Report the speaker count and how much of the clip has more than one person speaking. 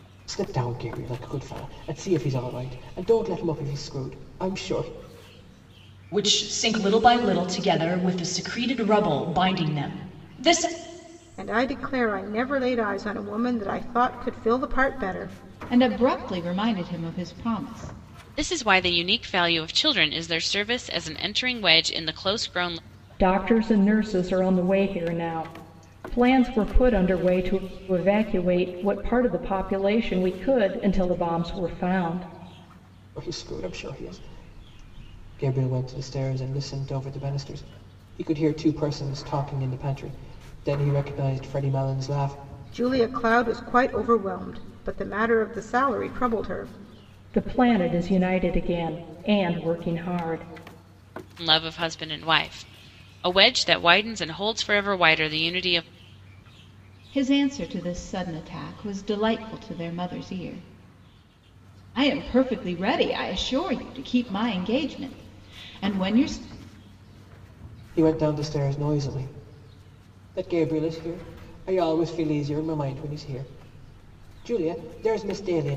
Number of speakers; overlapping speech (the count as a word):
six, no overlap